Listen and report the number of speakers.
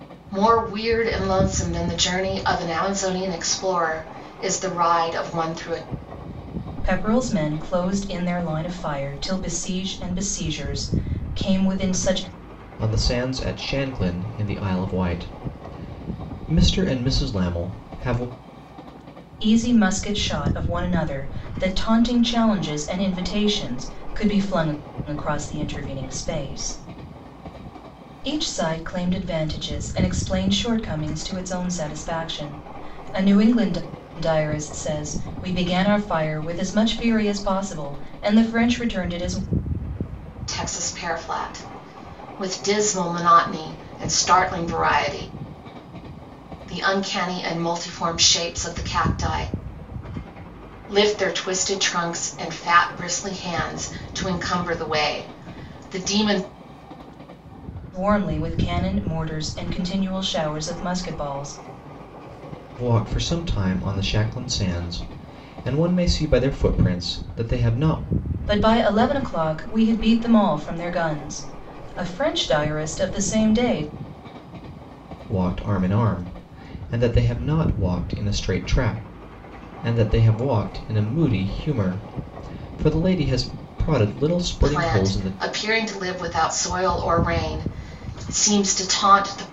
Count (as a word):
three